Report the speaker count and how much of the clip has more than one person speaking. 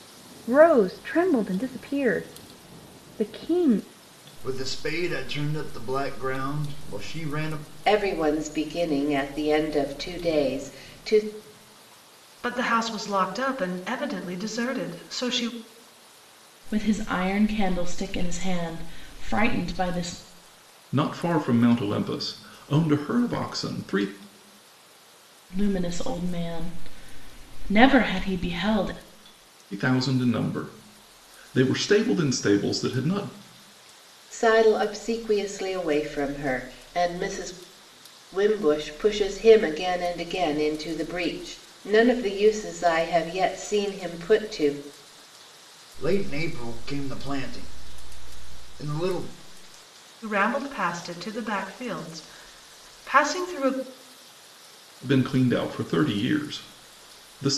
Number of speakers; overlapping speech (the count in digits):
6, no overlap